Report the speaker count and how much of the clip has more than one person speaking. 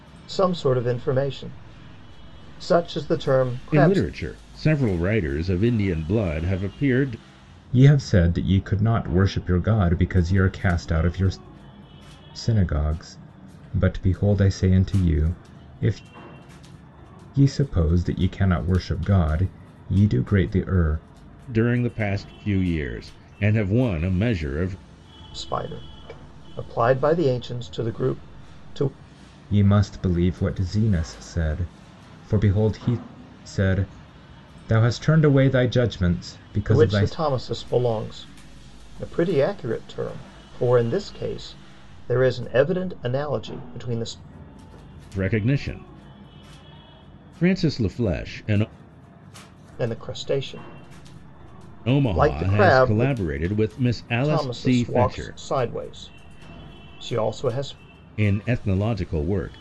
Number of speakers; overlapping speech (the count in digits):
3, about 6%